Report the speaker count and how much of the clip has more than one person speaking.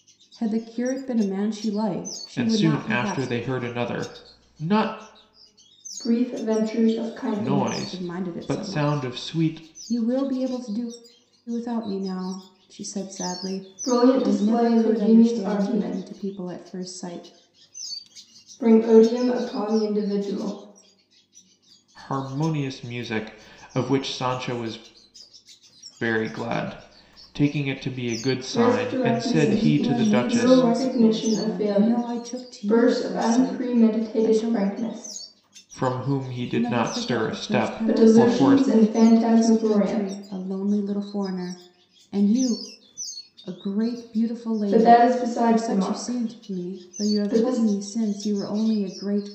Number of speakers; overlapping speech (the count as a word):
three, about 36%